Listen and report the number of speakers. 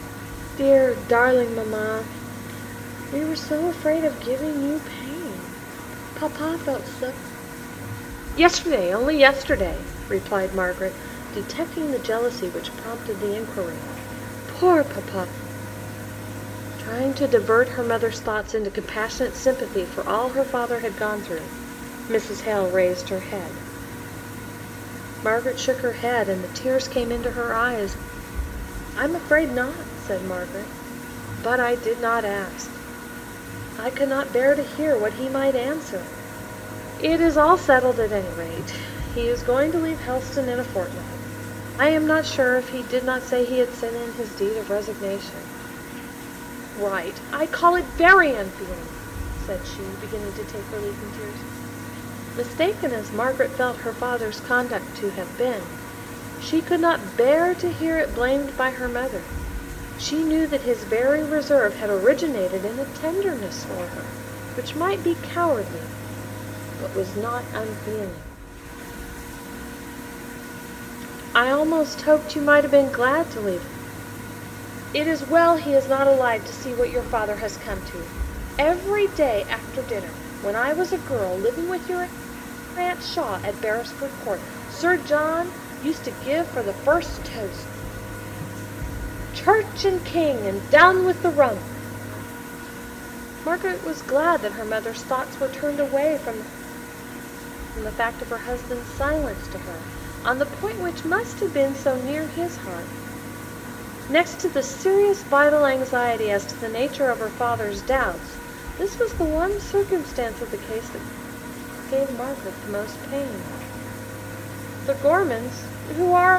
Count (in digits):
1